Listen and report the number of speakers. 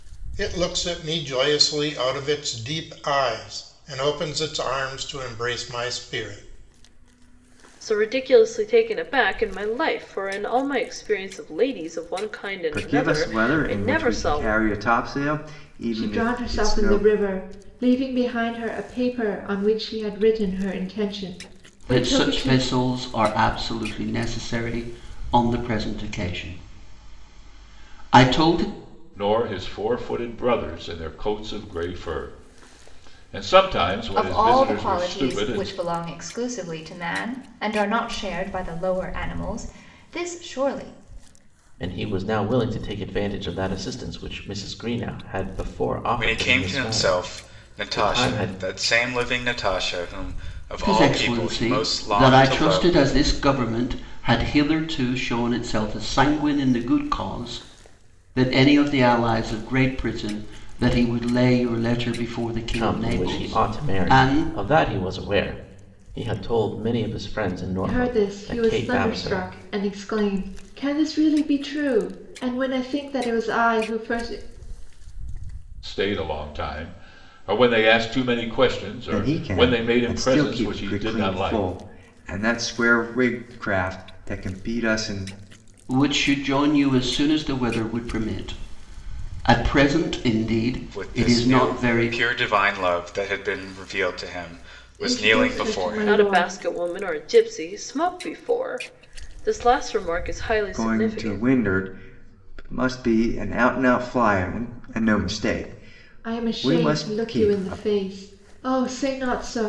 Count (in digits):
9